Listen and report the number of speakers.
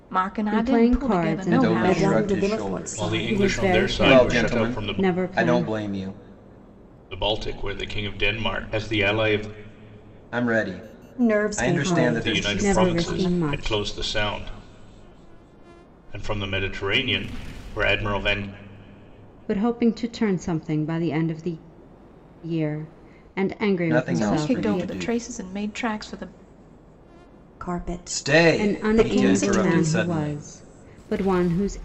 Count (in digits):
5